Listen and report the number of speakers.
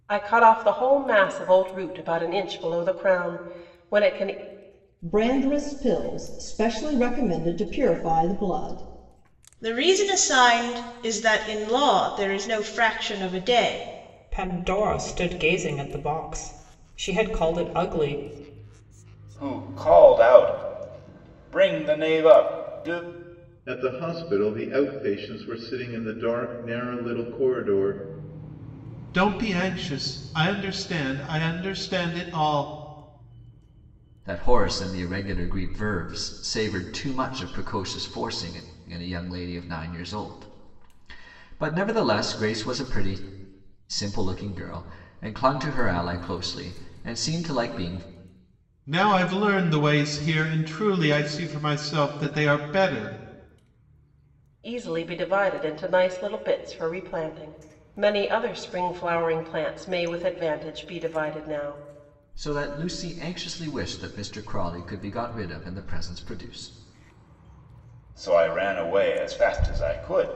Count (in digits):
8